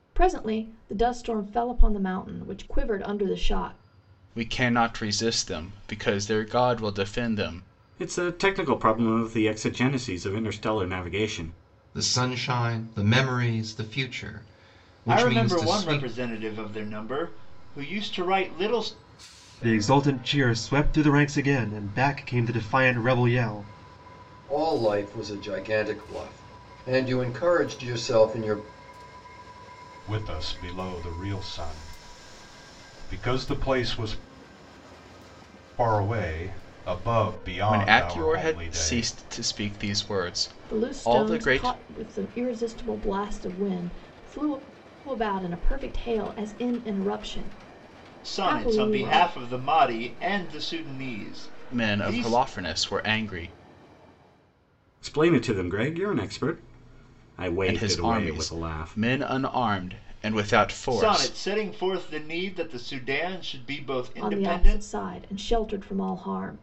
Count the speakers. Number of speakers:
8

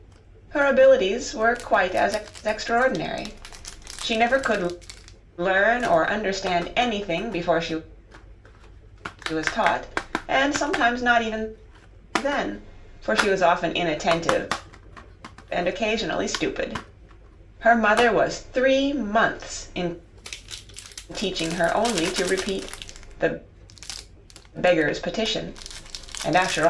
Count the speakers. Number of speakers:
1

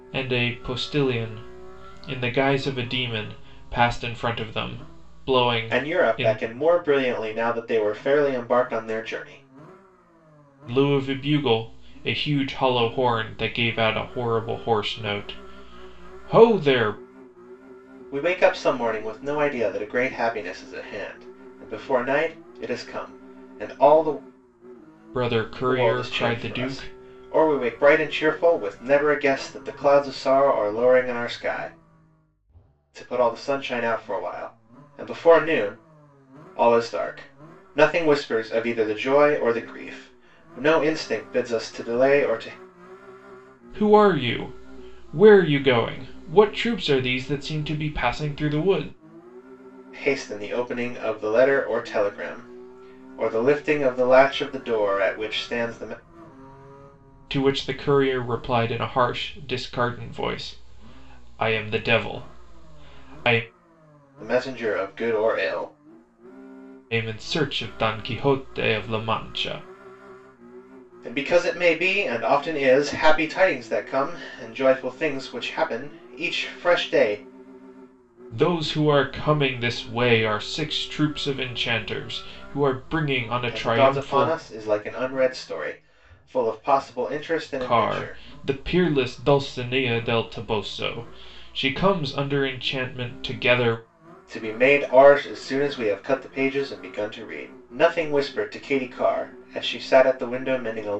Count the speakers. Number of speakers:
2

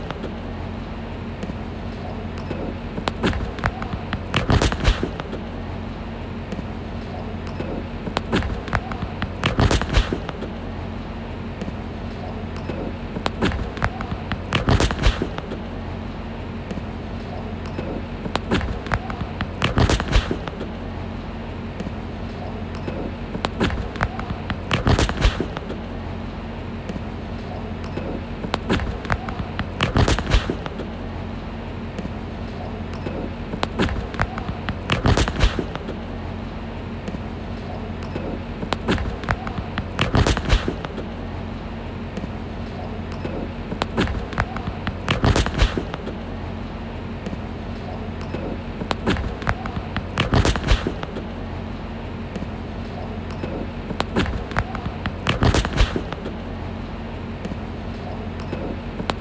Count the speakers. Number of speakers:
0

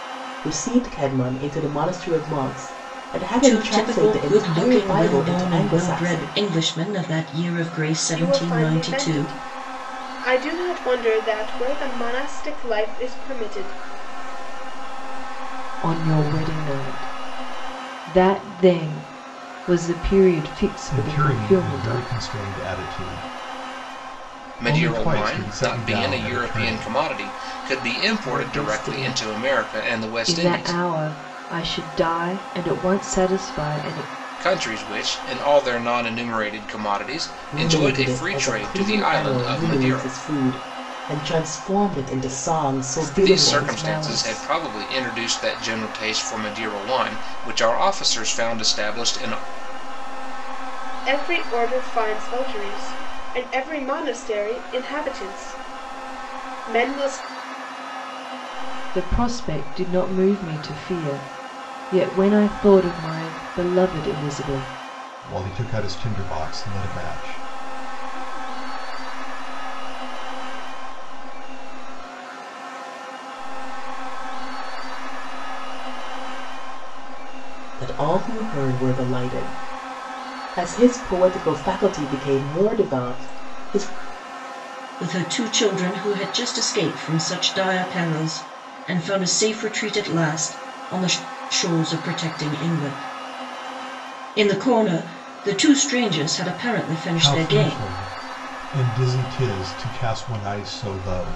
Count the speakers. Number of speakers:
7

